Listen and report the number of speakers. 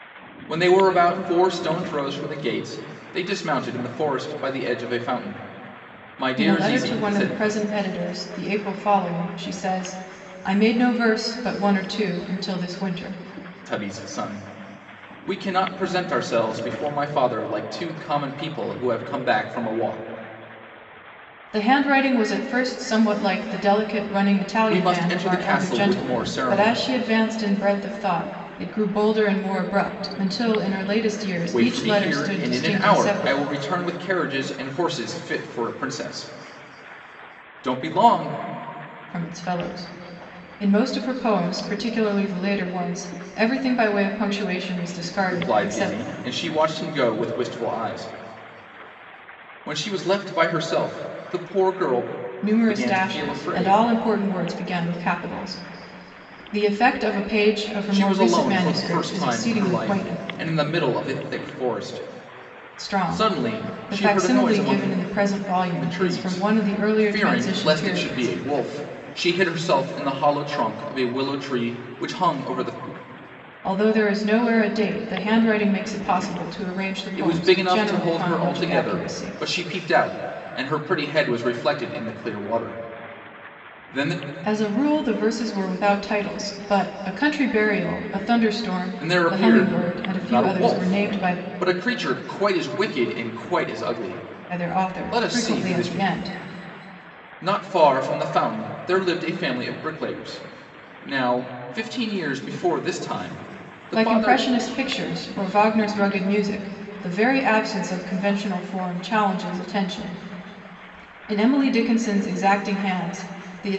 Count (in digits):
2